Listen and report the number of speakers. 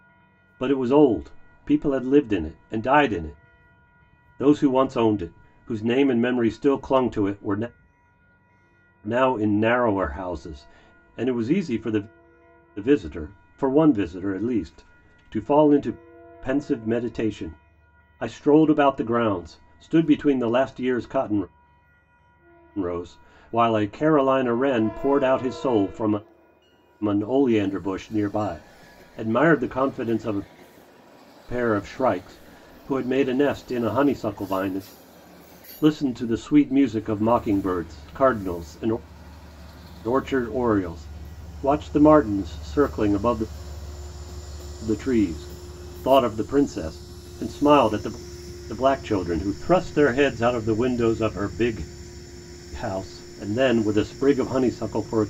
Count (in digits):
1